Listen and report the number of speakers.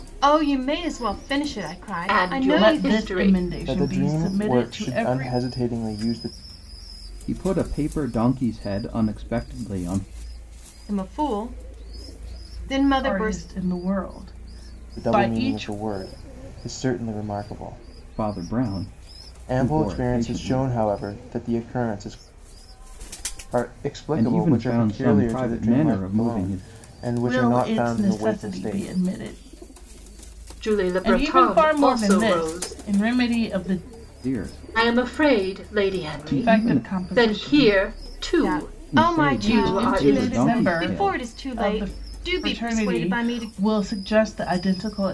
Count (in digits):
5